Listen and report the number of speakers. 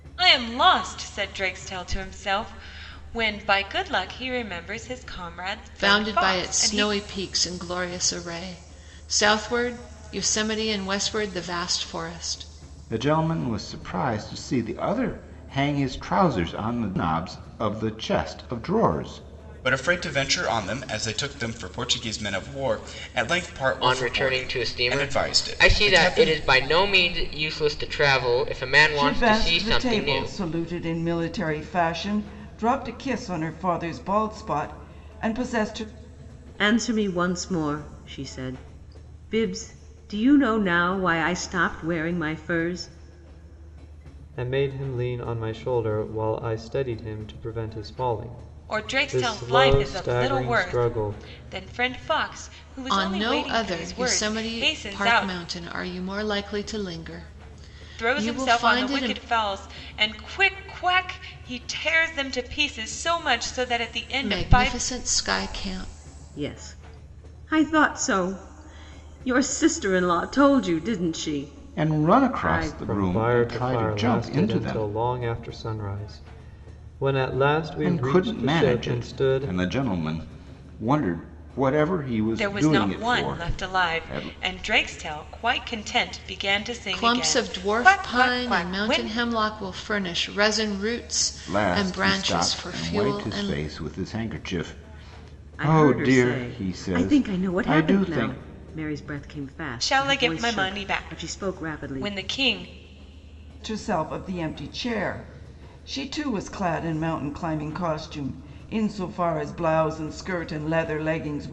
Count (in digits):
8